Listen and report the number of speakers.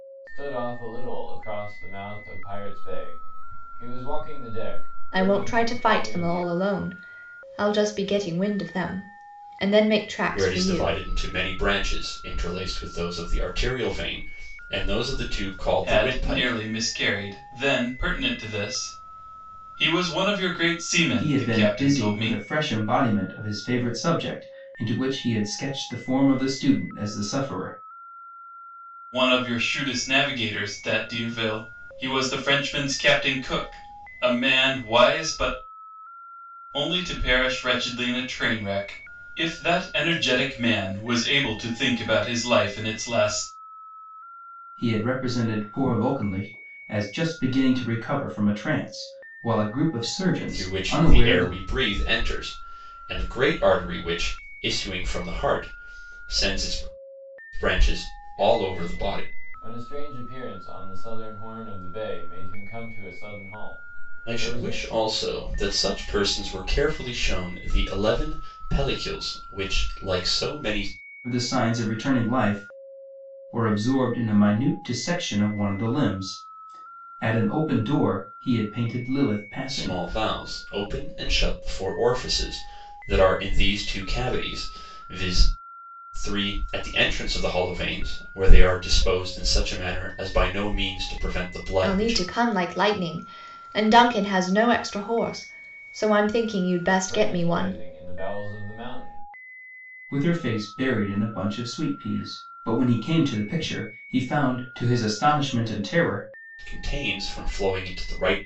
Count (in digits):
5